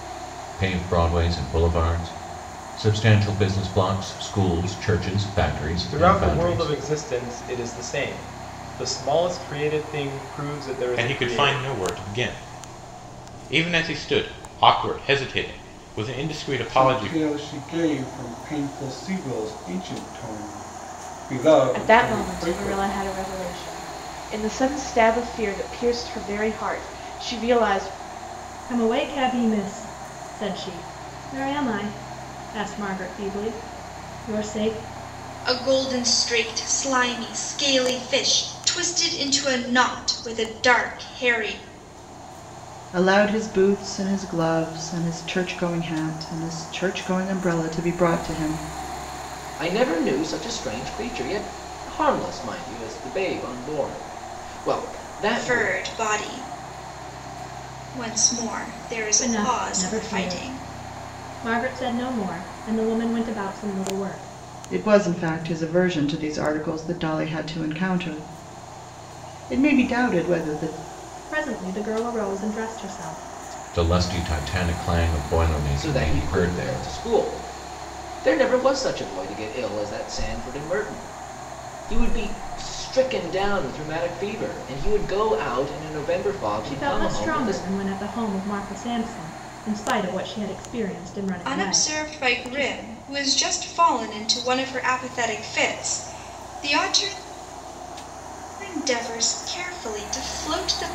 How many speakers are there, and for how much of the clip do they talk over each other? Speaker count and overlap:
9, about 9%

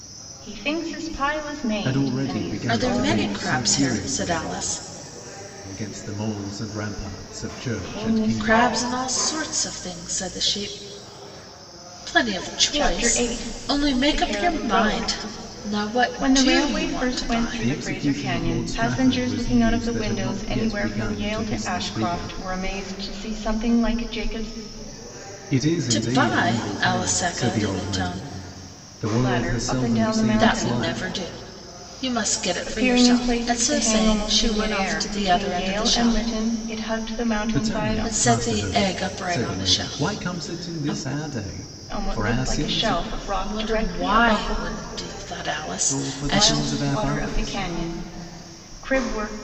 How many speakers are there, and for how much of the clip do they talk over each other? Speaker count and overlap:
3, about 57%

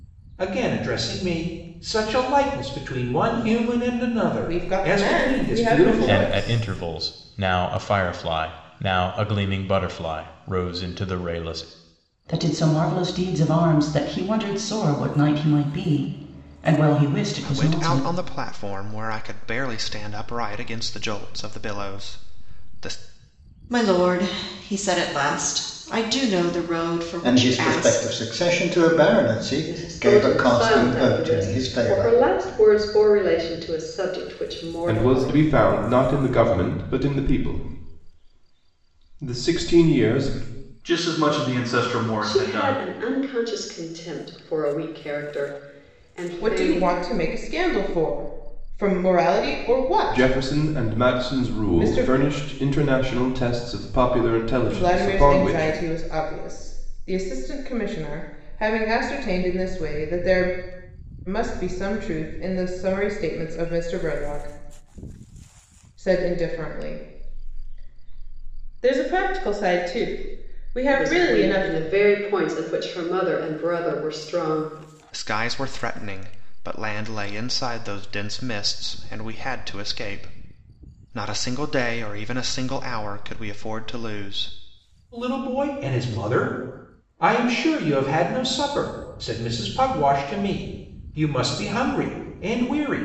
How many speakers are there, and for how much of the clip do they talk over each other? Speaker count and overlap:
10, about 14%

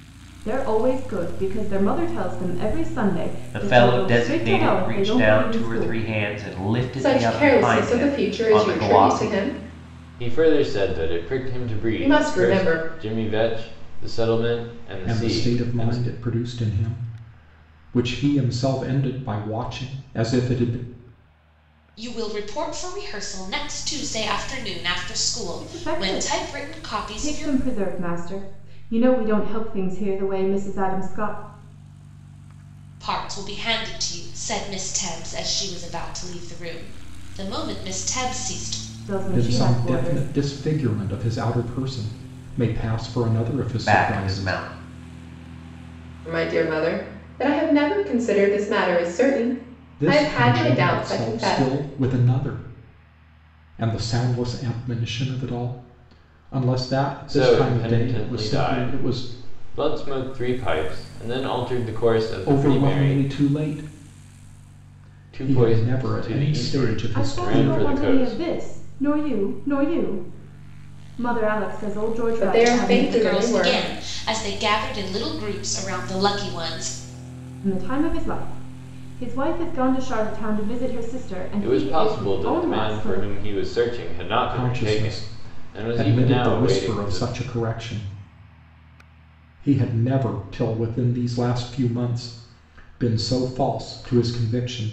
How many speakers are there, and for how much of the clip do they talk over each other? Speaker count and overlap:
6, about 28%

